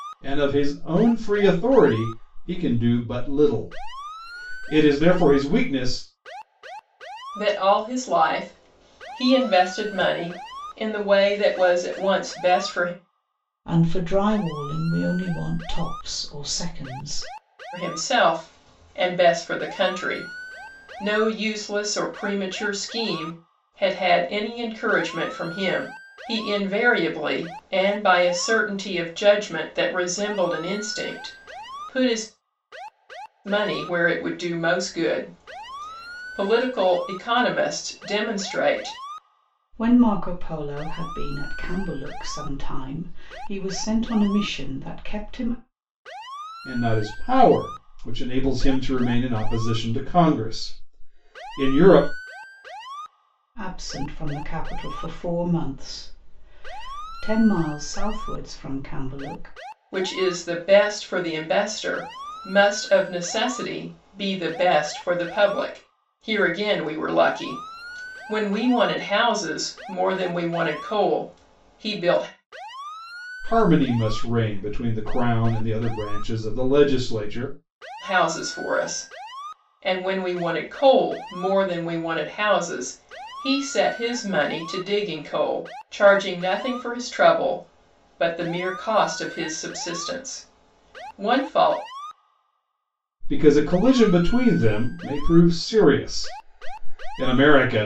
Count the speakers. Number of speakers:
3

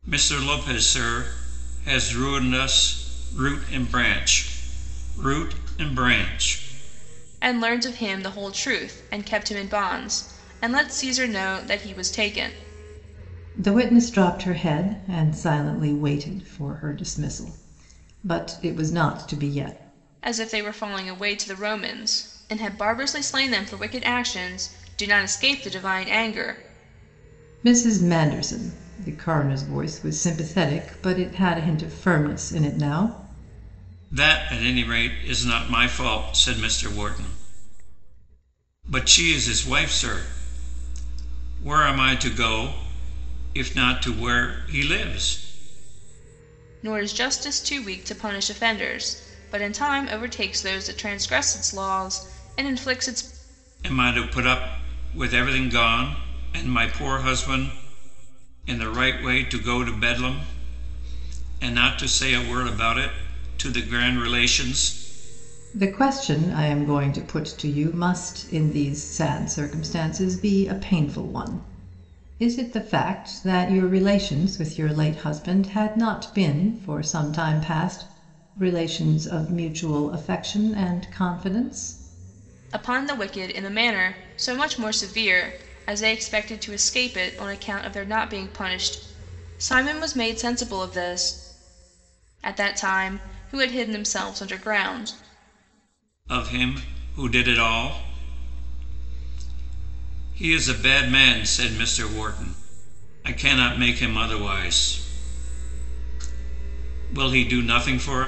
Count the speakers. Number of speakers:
3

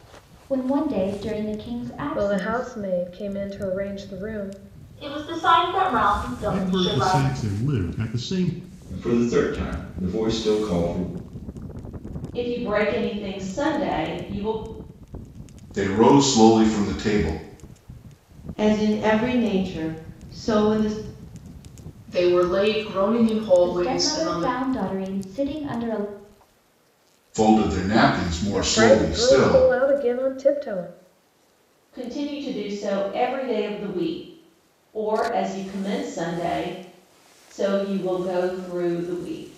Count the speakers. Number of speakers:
9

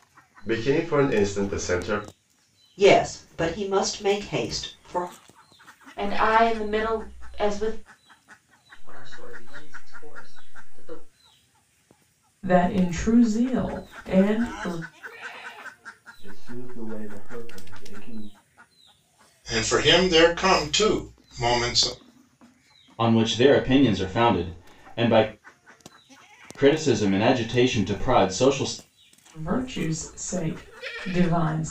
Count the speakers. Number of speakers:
8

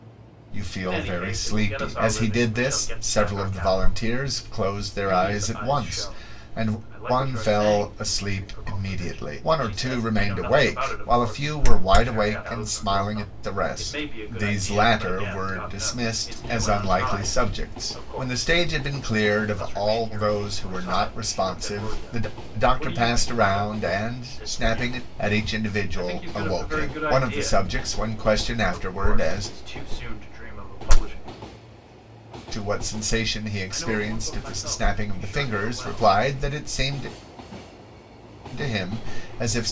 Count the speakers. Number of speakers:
2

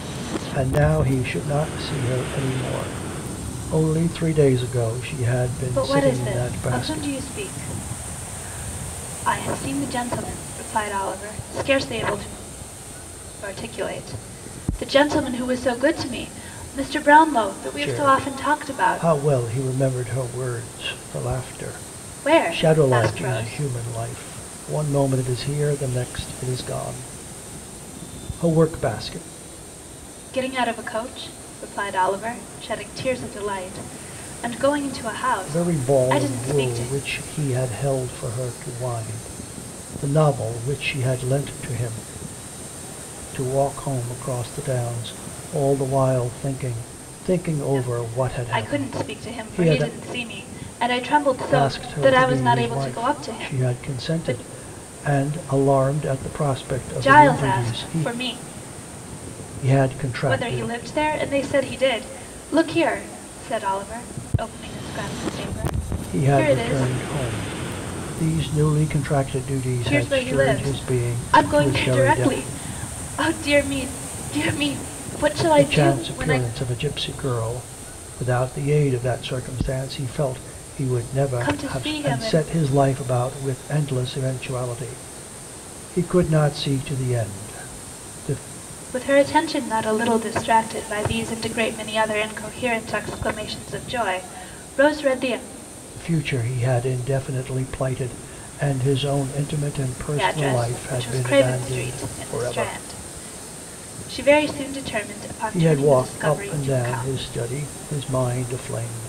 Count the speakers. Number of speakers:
2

